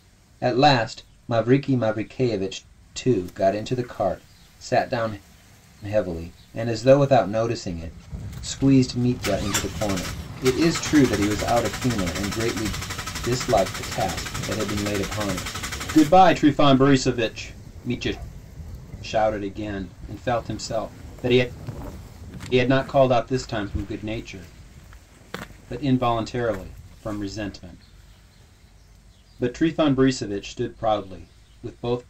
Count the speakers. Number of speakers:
1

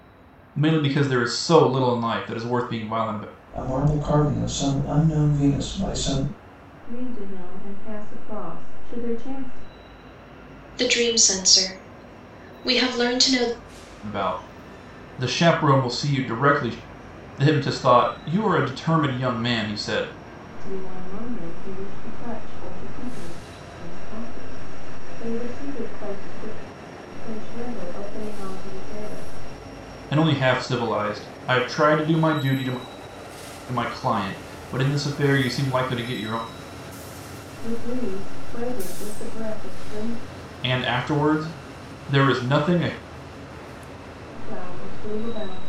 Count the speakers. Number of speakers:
4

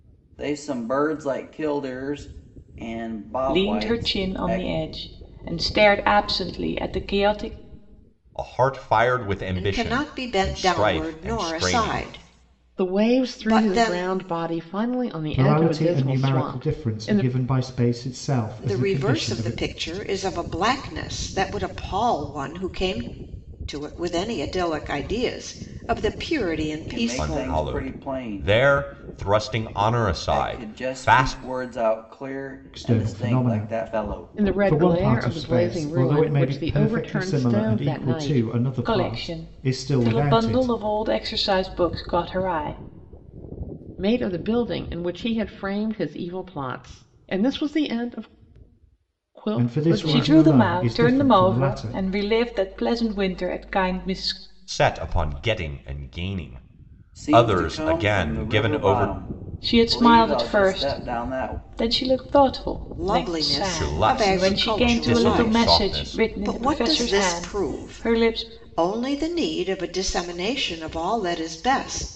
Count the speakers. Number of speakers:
6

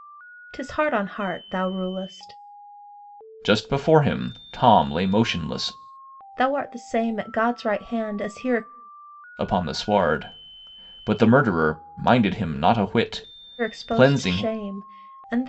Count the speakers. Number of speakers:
2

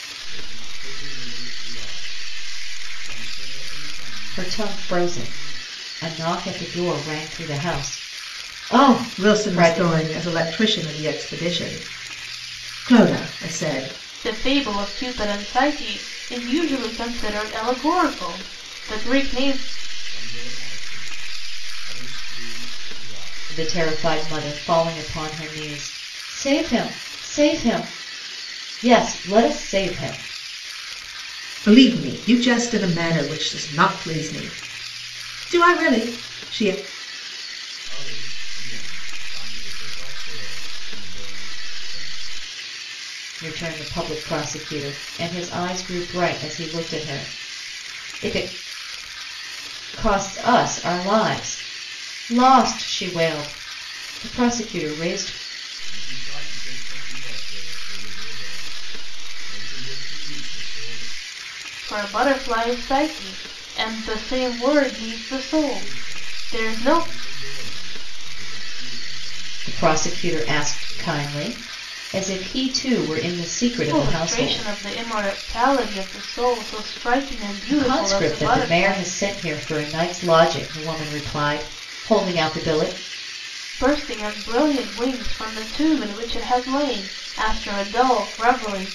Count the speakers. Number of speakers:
4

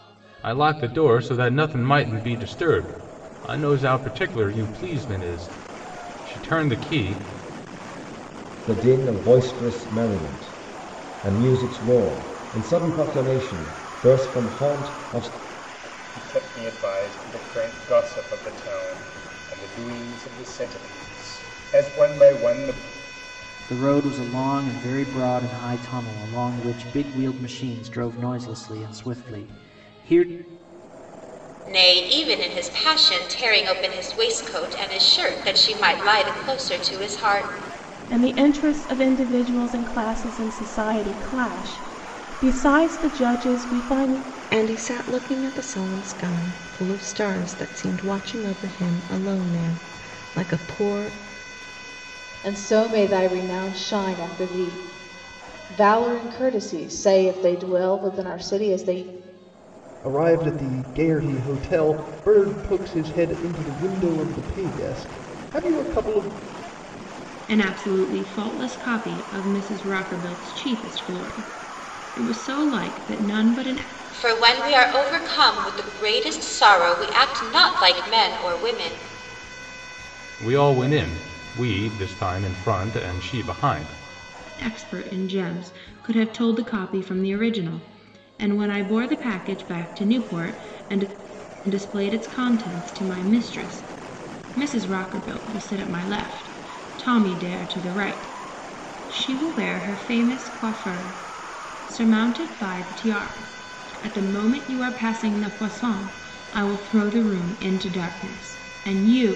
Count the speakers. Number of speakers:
10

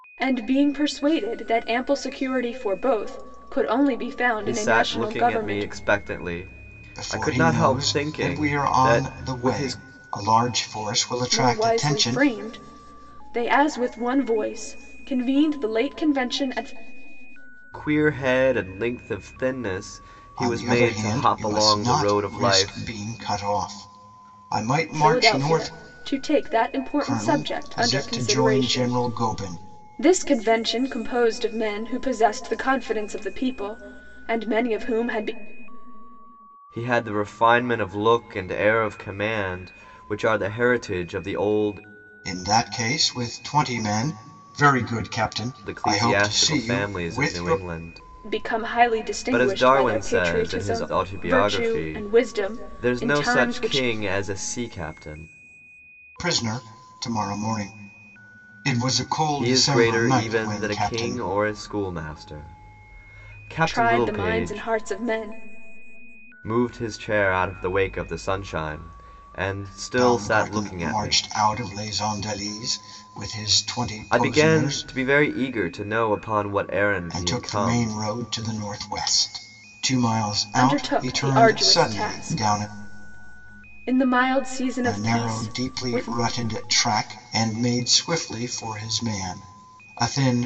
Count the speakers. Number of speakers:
3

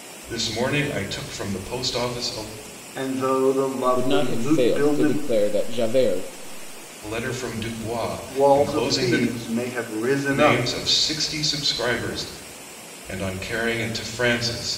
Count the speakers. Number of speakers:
3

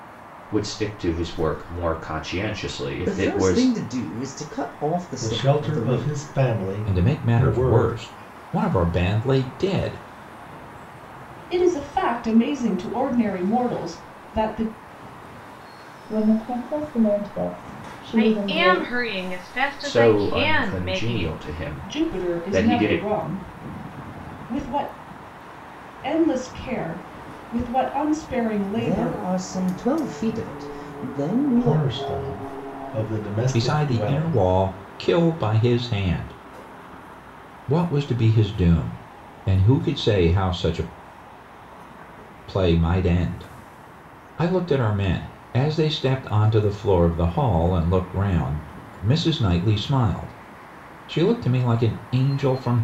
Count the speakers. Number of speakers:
7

